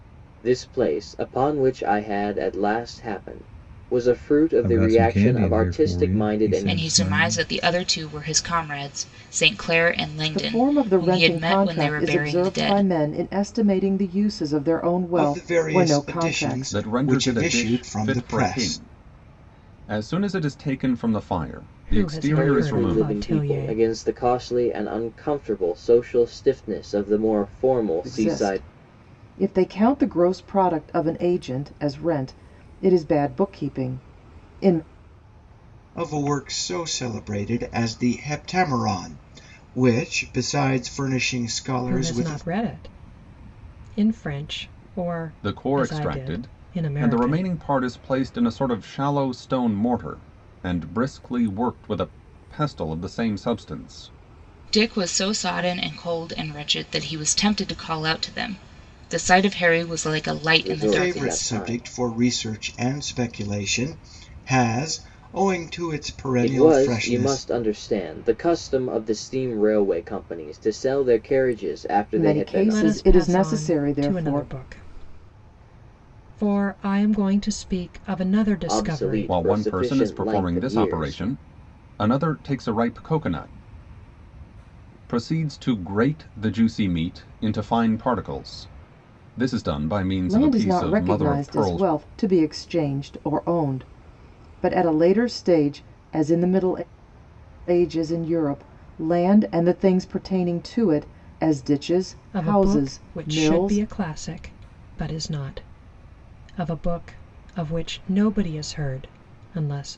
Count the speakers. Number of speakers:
seven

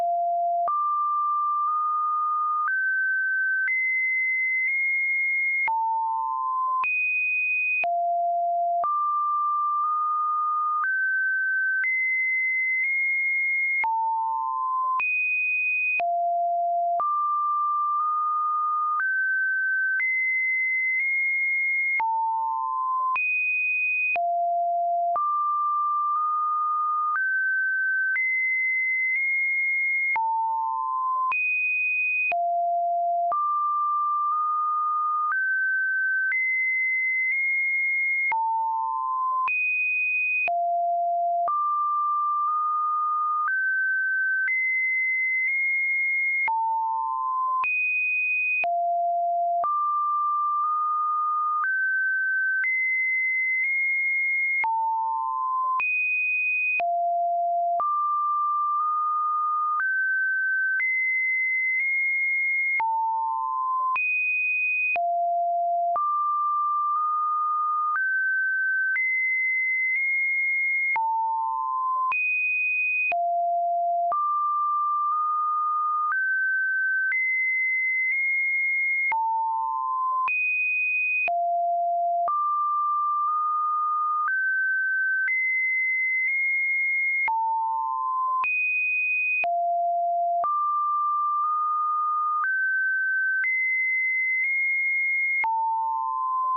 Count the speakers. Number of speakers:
zero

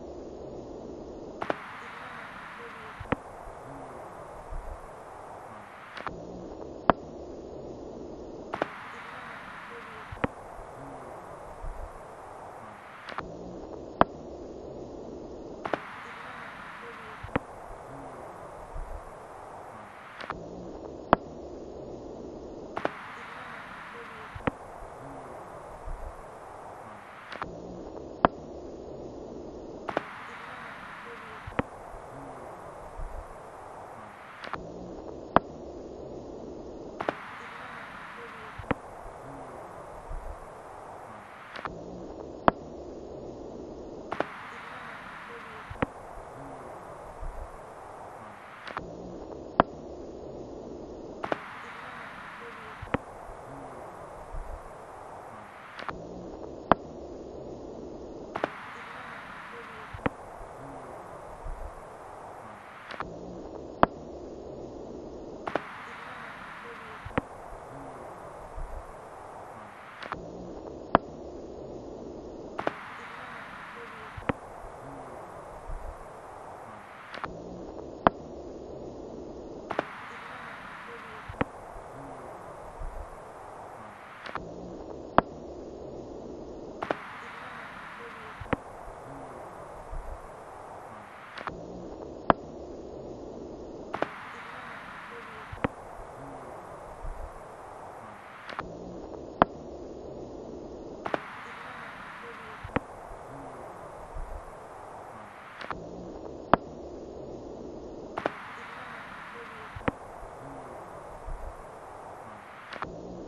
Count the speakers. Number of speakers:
zero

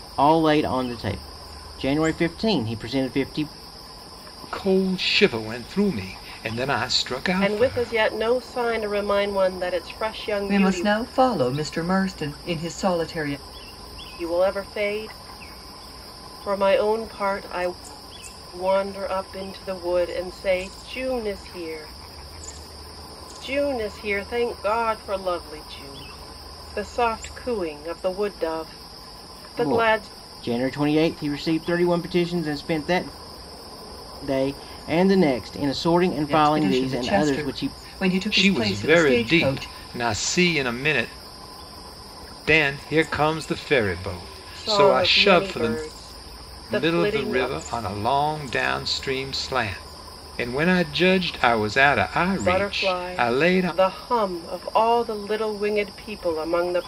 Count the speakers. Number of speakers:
four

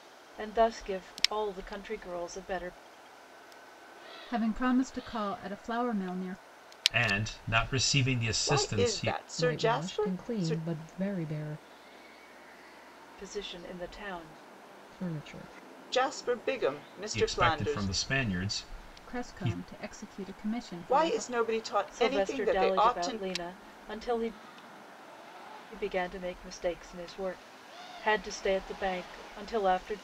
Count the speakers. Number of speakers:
five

